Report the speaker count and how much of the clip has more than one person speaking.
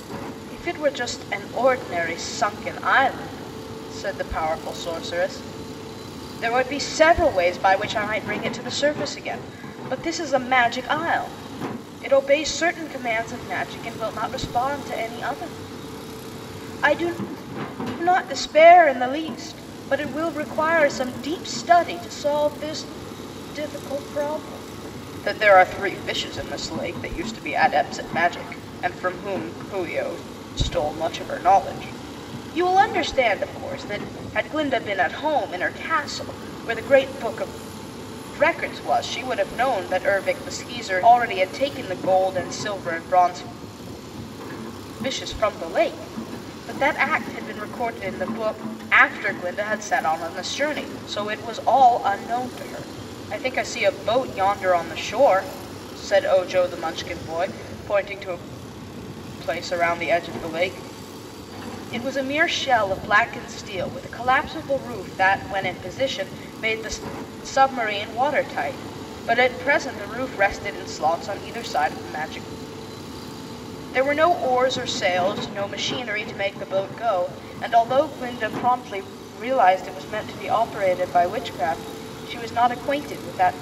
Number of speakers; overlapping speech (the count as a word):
one, no overlap